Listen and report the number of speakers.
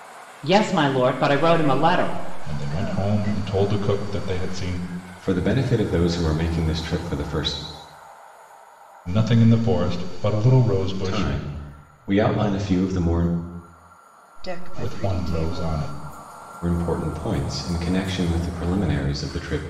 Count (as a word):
four